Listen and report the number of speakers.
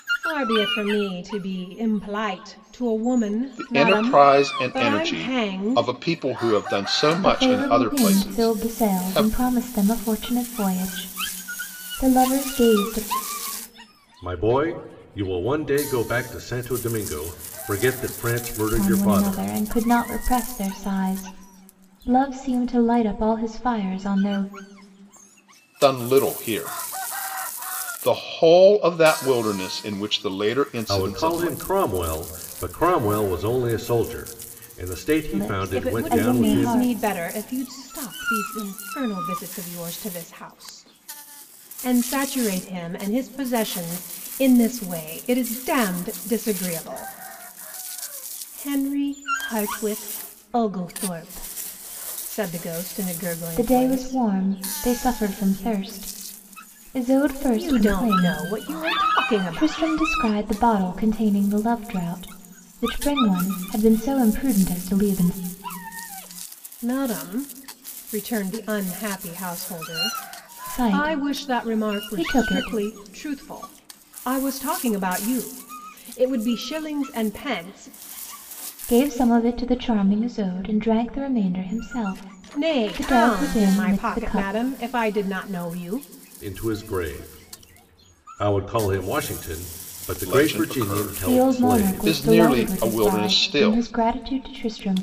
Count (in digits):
4